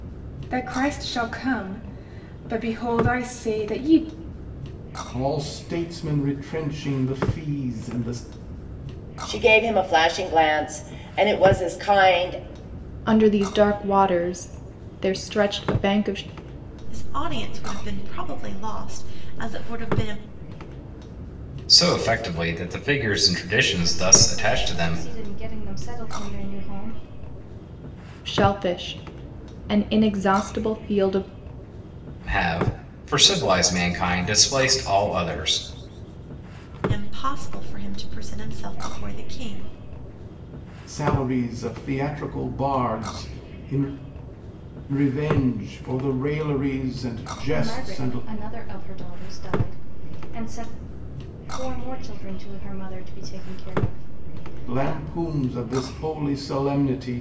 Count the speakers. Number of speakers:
7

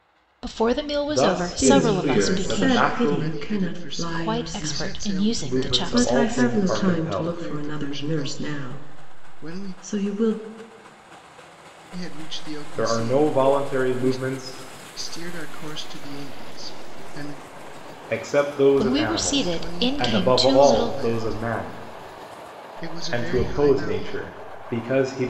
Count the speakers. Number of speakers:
4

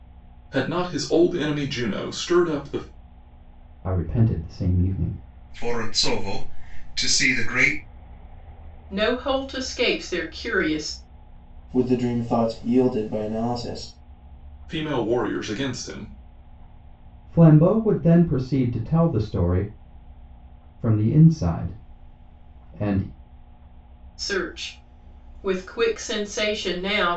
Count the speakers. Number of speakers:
5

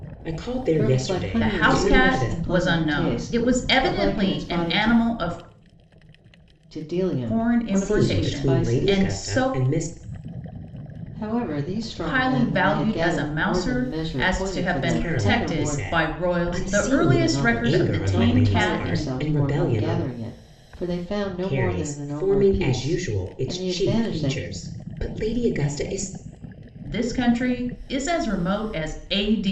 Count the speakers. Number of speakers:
3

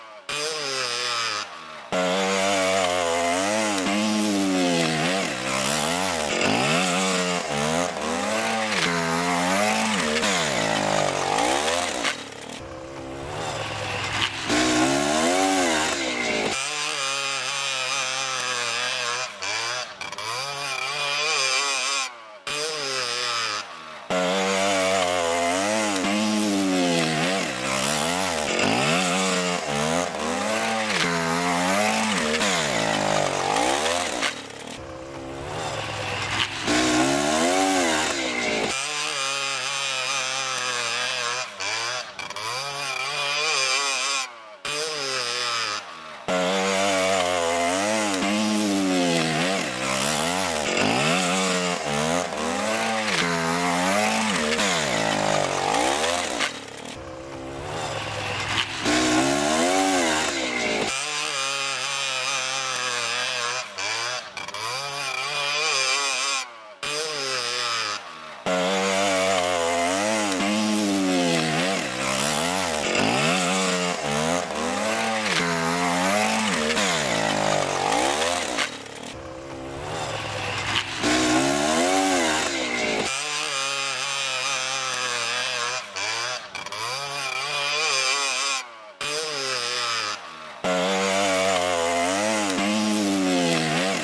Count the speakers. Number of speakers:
0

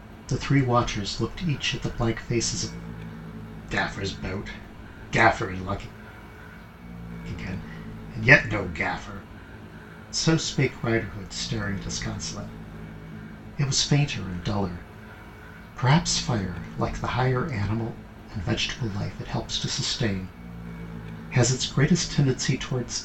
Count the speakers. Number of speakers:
1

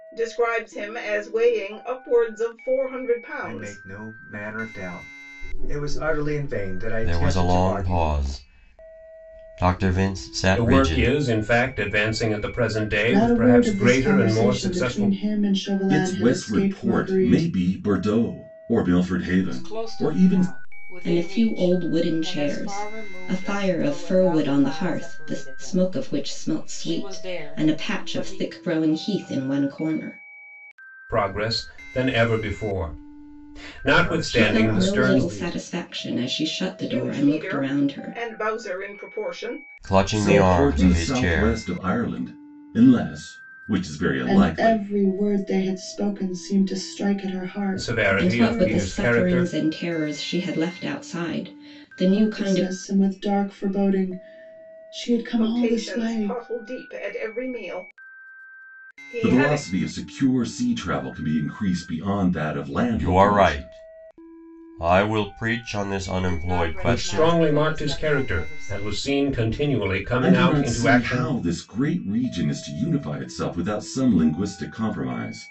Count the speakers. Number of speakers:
8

